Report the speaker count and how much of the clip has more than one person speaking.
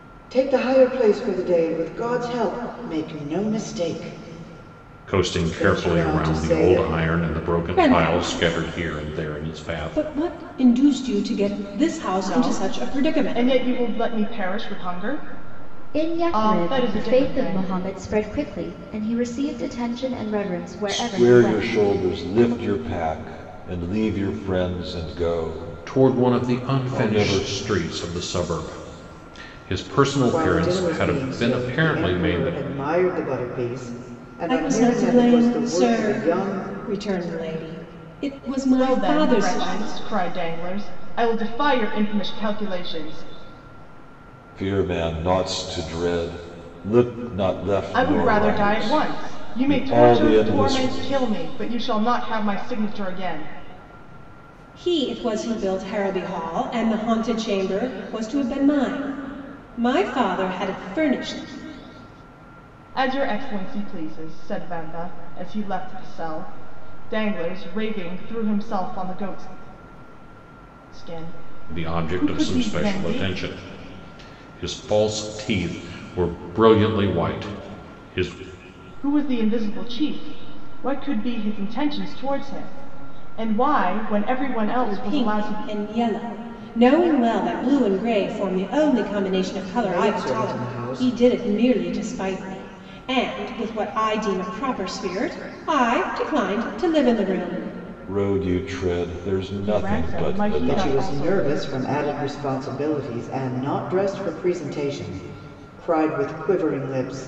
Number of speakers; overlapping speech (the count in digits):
6, about 23%